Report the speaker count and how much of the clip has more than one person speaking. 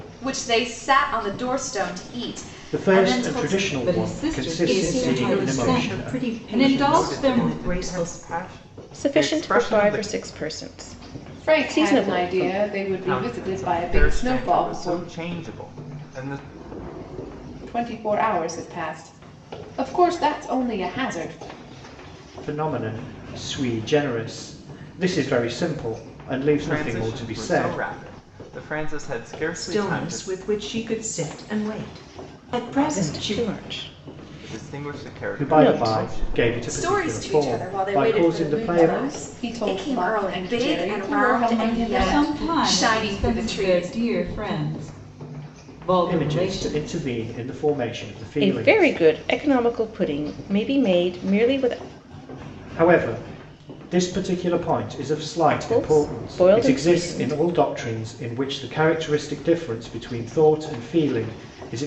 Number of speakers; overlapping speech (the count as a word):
seven, about 41%